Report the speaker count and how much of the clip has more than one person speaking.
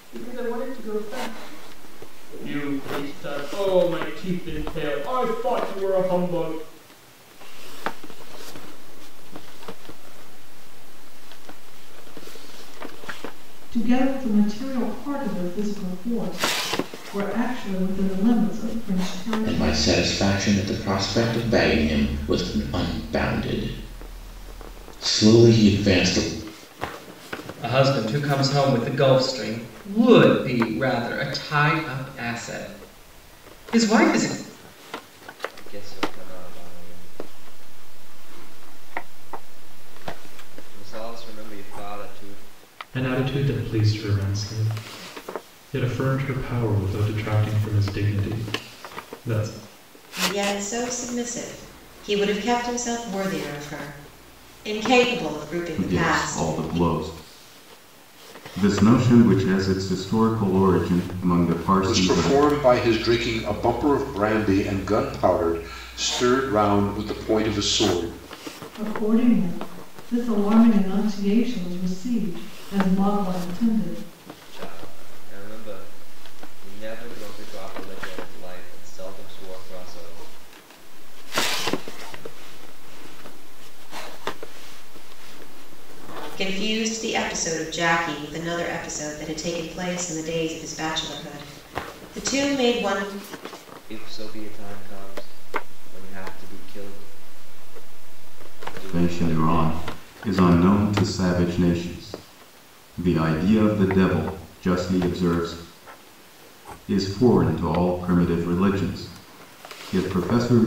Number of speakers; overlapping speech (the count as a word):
ten, about 4%